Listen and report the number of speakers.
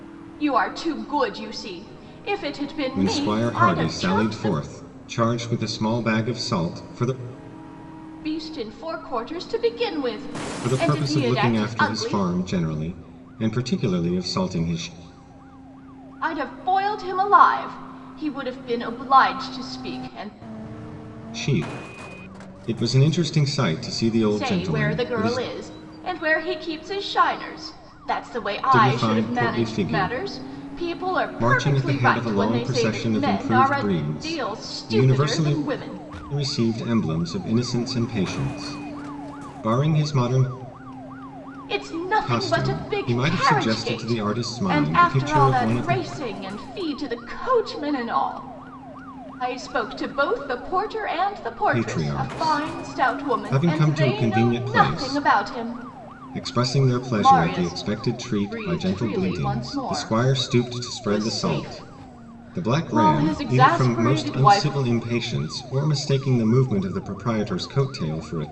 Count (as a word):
two